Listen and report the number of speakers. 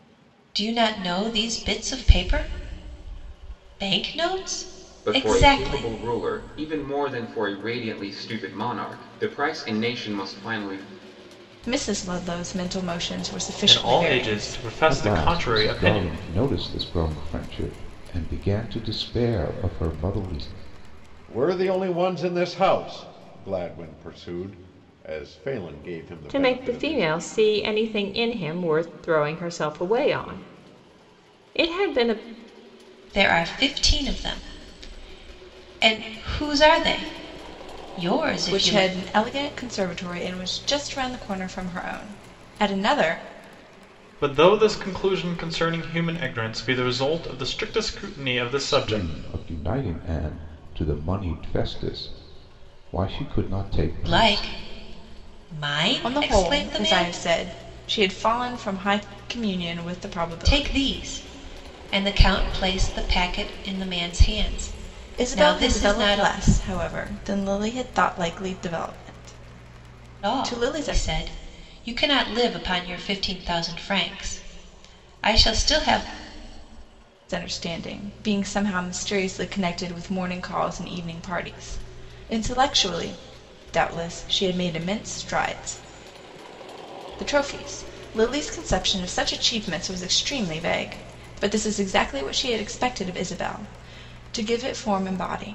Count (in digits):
7